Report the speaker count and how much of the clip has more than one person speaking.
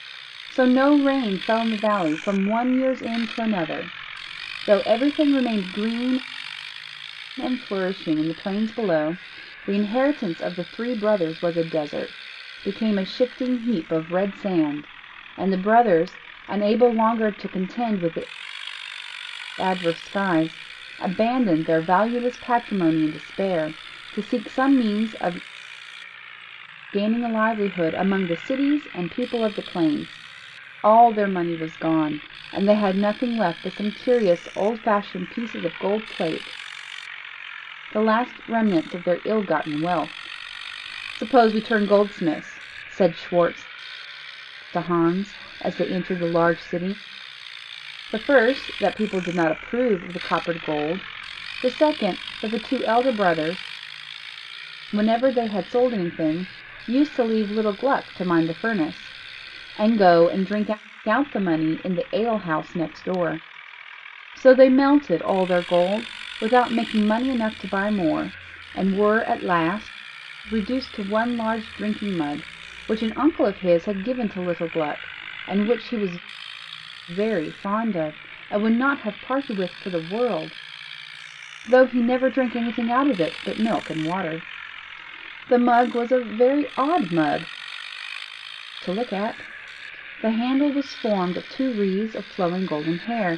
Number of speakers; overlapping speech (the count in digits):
1, no overlap